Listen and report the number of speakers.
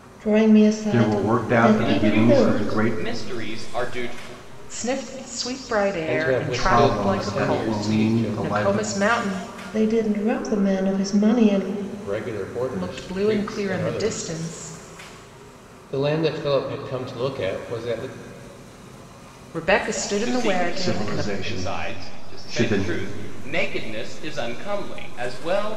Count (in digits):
5